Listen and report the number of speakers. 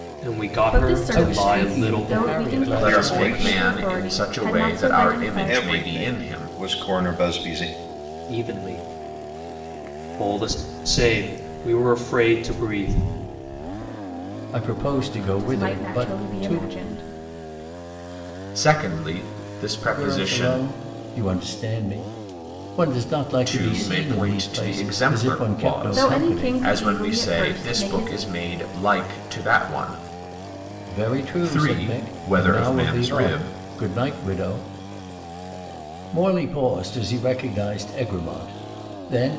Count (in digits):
5